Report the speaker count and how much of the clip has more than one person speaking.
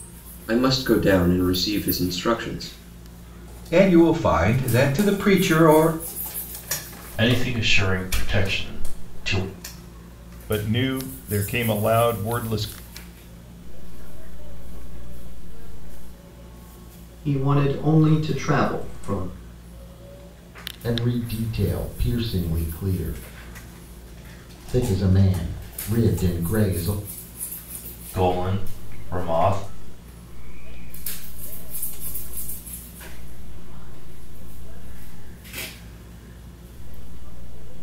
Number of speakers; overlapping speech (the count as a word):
seven, about 3%